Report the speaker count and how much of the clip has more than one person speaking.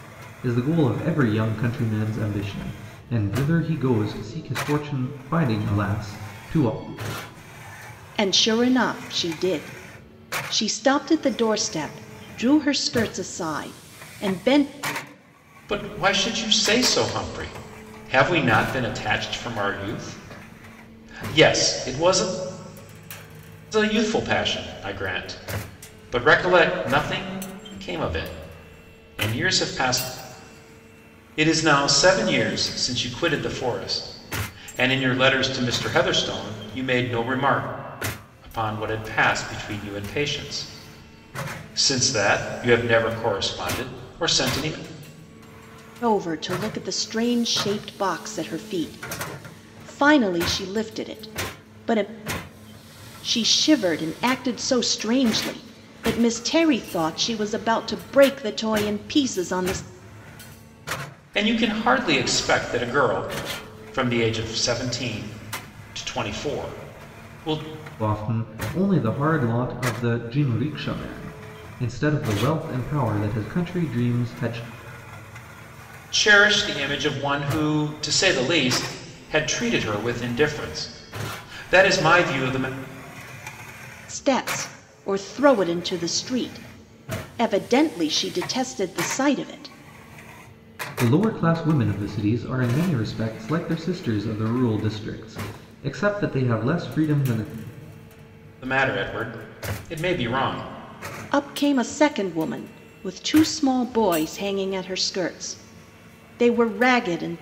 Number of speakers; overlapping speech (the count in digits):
3, no overlap